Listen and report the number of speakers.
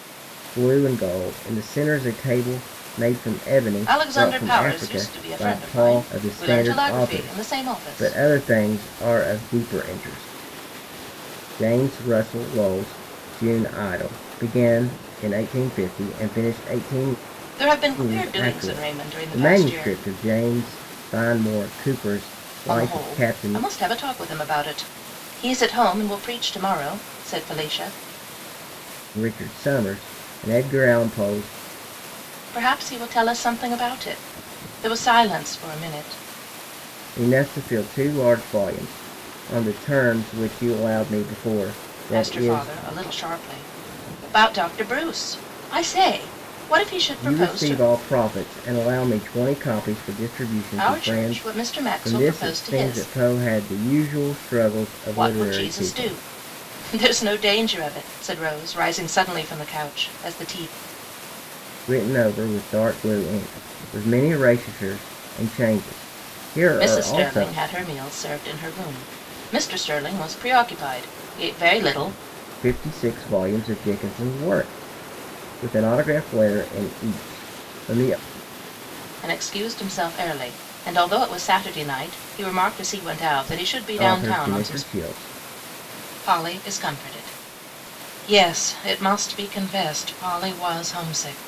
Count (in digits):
2